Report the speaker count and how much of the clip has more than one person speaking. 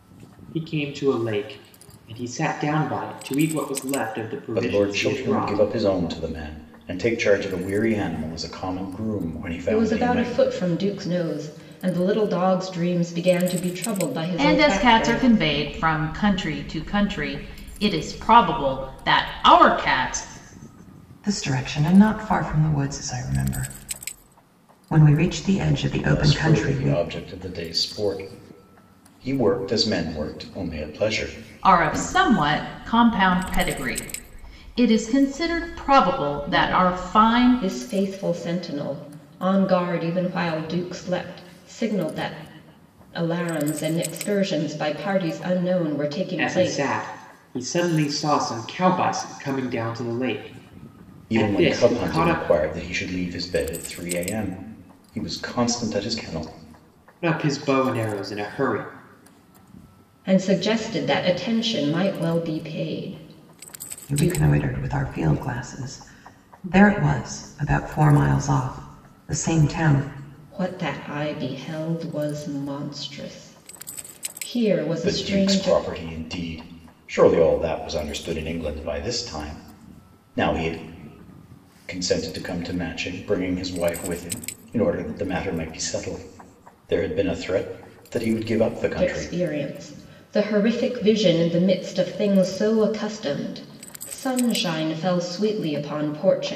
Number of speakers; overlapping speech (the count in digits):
5, about 9%